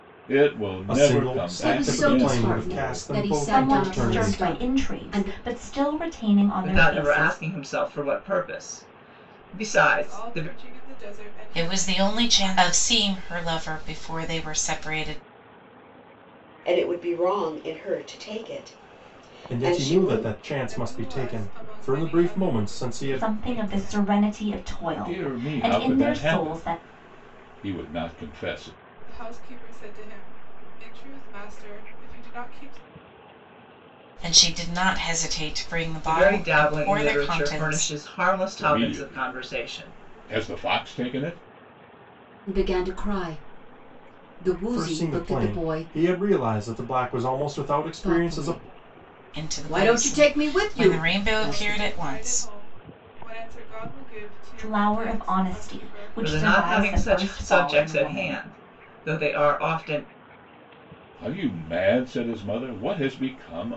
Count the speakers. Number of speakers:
8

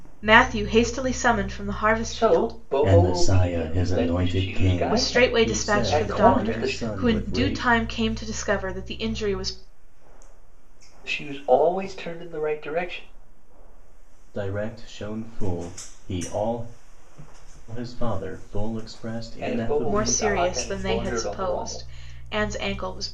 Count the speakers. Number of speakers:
3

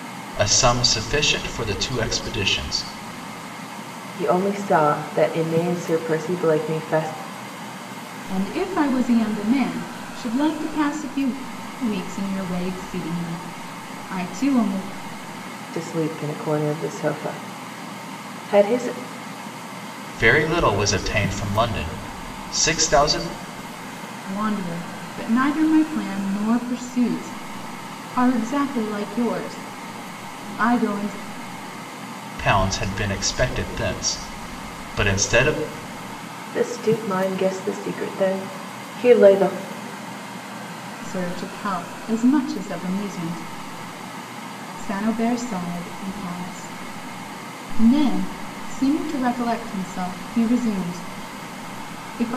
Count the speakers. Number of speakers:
3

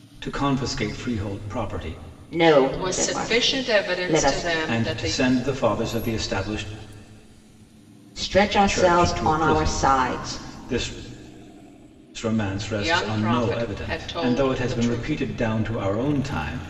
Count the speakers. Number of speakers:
3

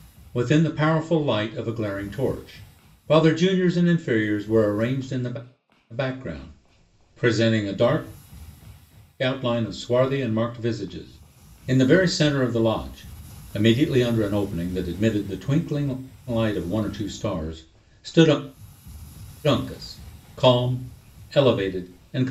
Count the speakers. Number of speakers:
1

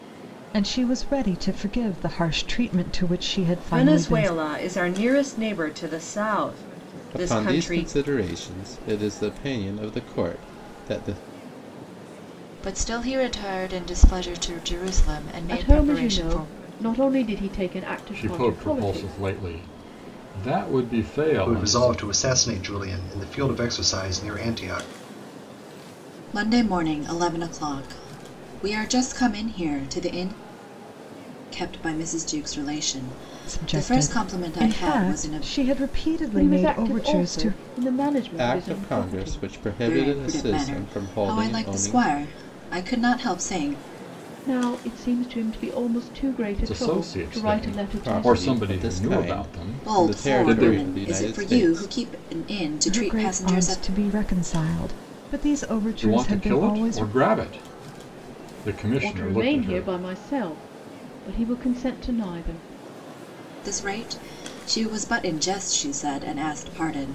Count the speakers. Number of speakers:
7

